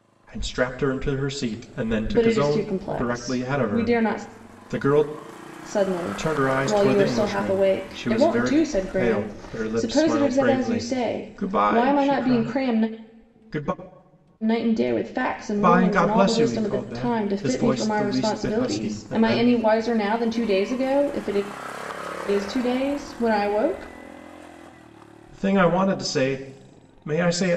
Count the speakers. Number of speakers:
two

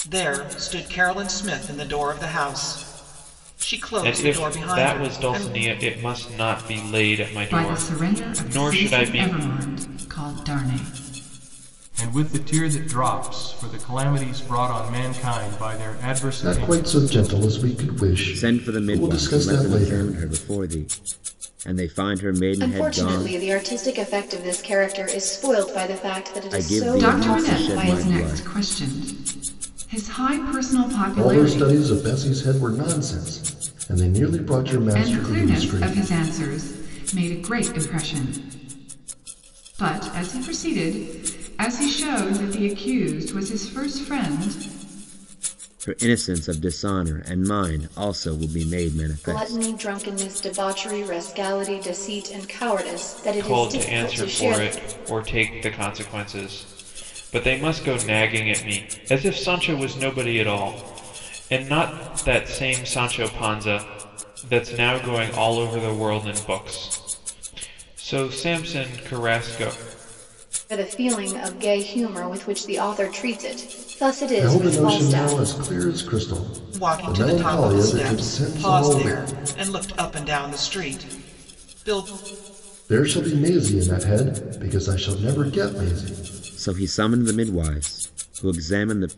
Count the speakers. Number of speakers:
seven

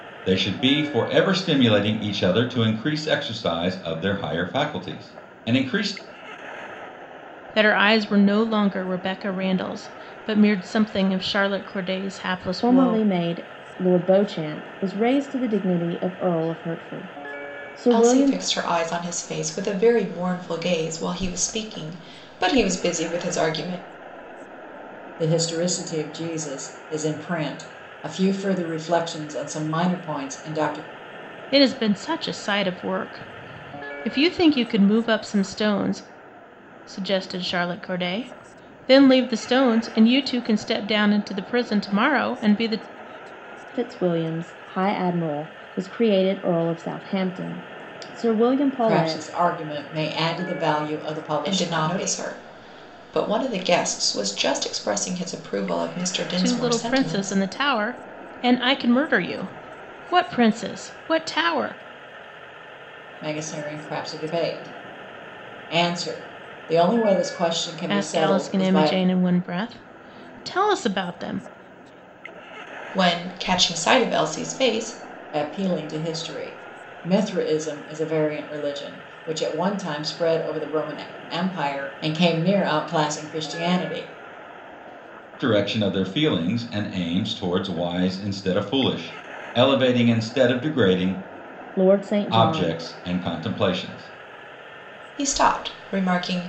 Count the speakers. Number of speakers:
five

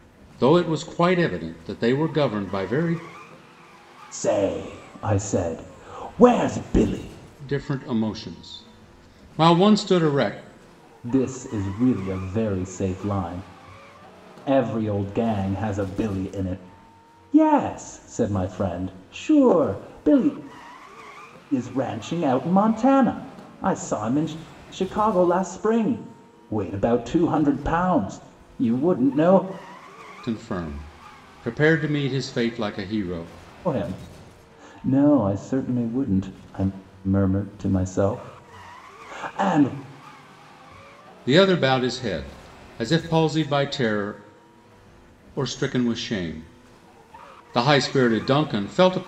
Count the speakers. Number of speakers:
two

